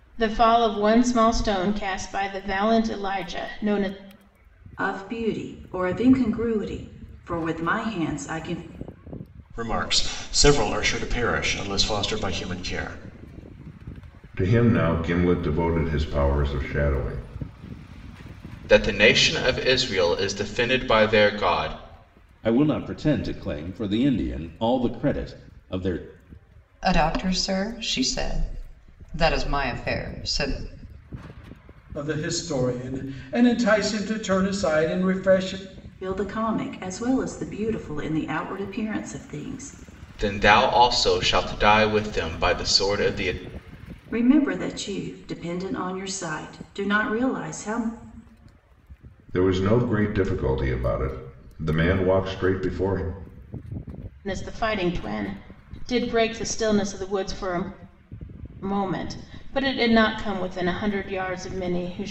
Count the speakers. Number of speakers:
8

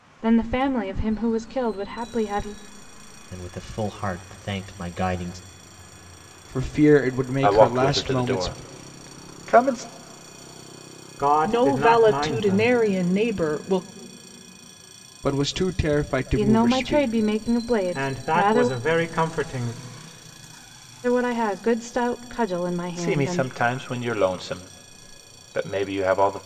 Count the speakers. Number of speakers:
6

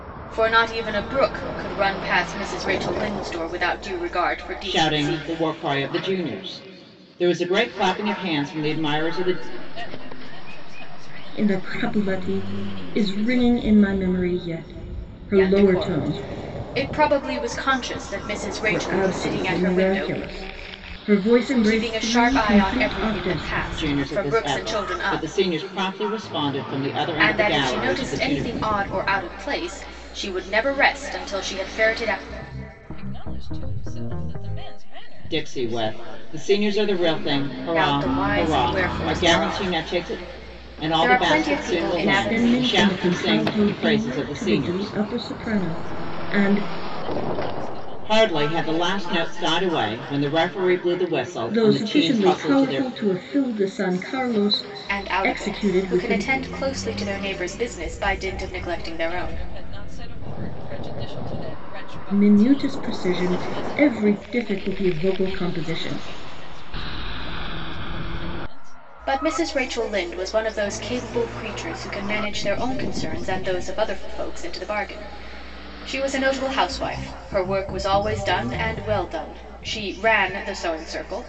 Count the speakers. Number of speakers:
4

